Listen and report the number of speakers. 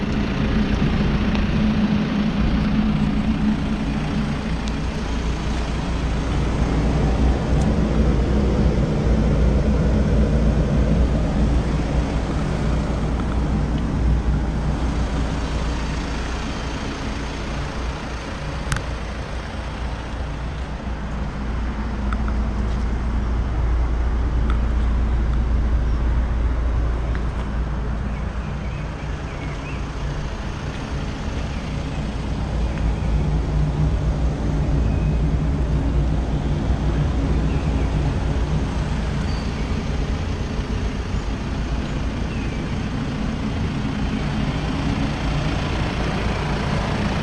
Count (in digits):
0